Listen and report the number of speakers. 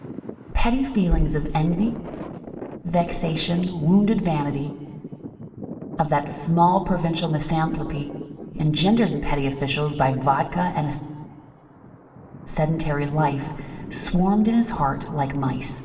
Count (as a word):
one